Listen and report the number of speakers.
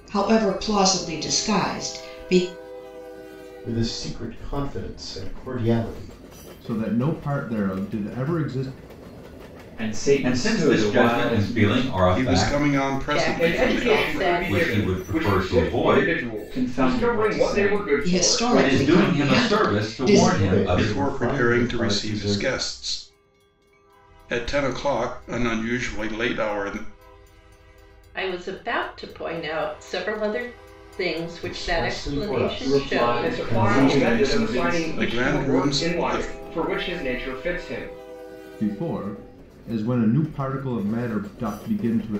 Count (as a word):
eight